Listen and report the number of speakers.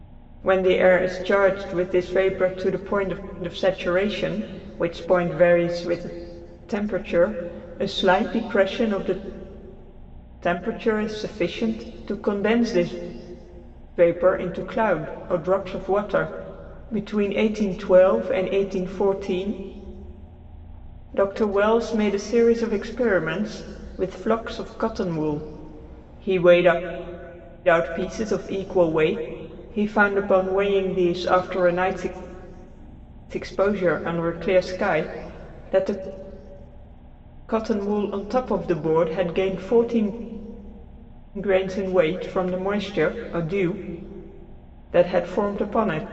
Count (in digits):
1